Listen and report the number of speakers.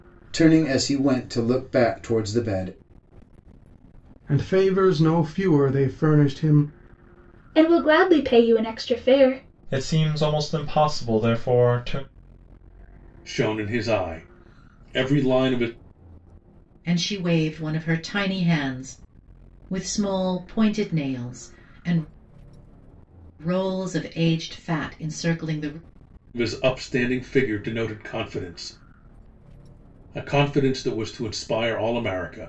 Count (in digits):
6